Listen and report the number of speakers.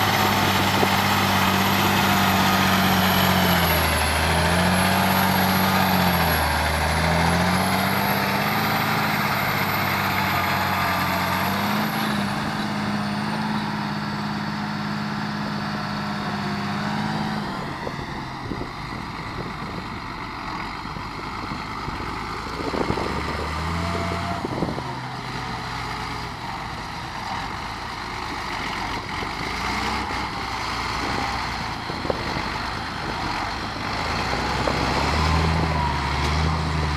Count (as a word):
zero